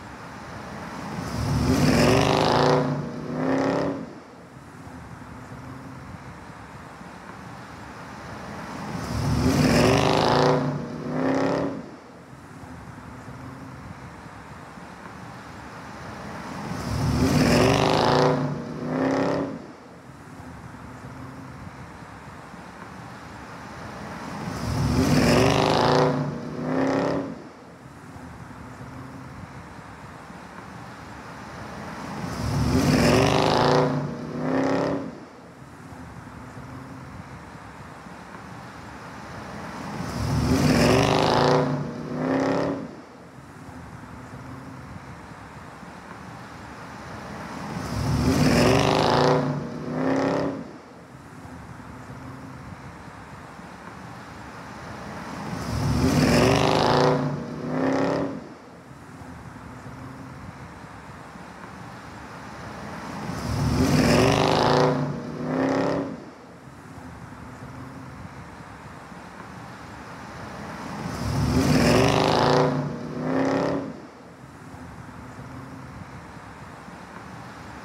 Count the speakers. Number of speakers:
0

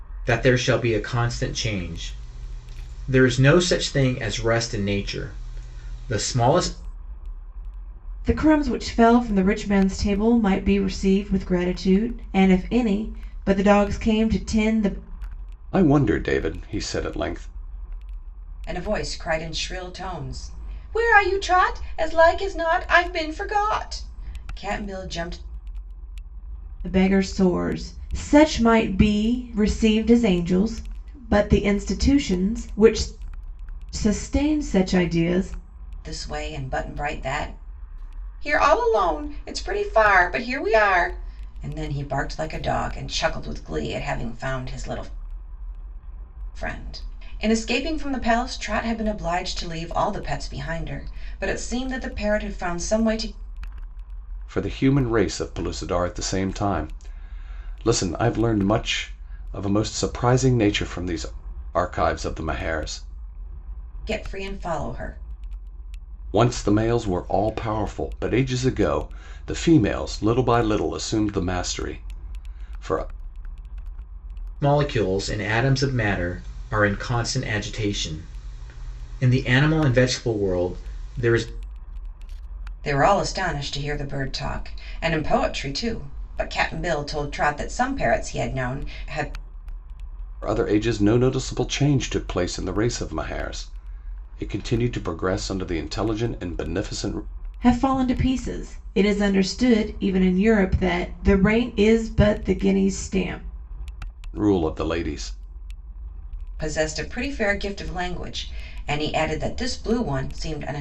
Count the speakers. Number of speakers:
4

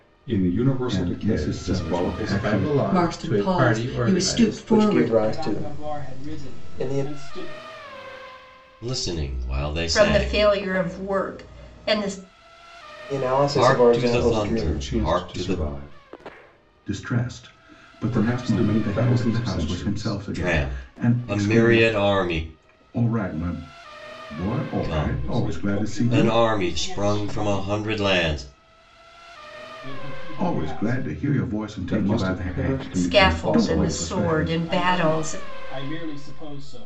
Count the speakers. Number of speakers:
8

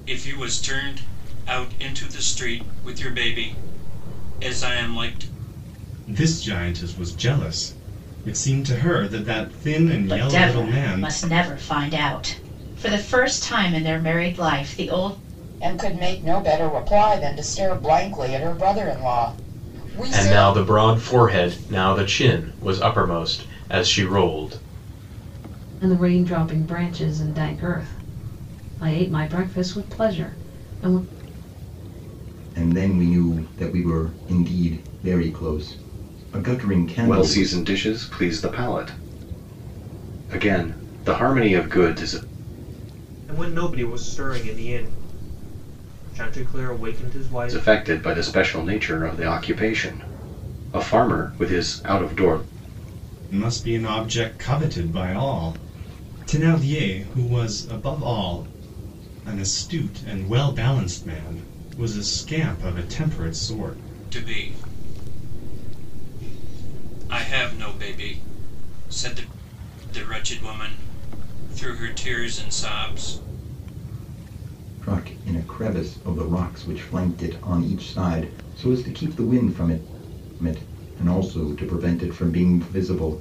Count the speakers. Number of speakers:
9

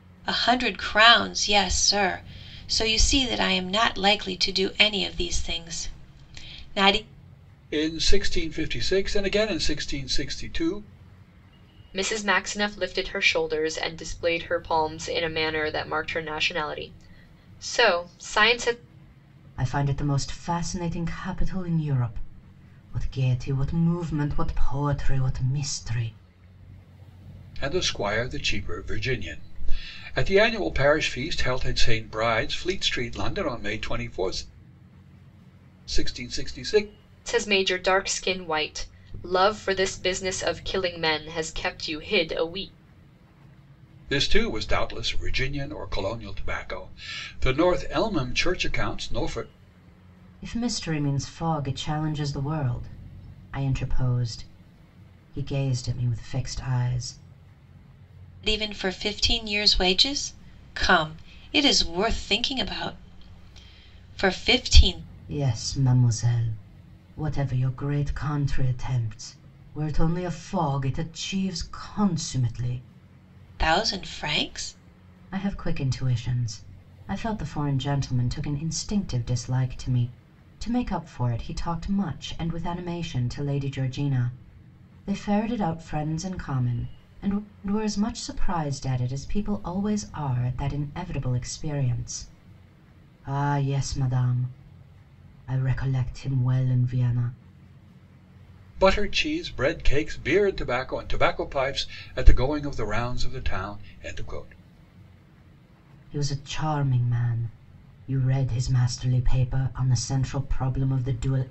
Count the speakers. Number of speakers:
4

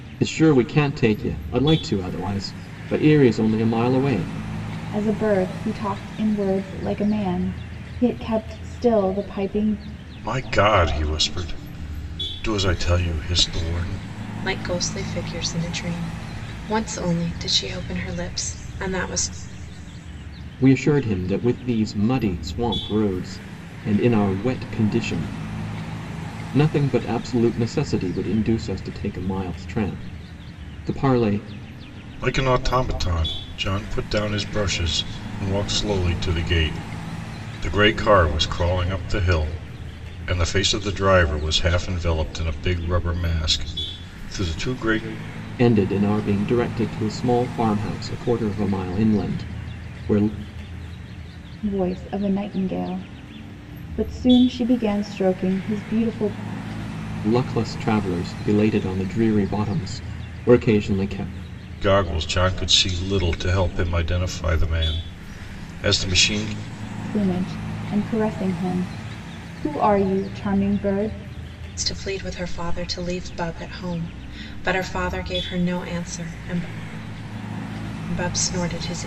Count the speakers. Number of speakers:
4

